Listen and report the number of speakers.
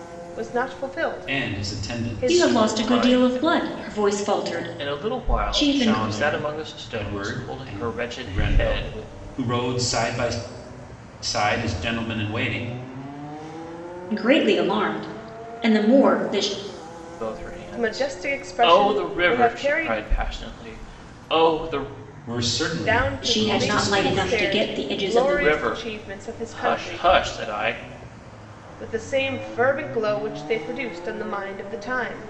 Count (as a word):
four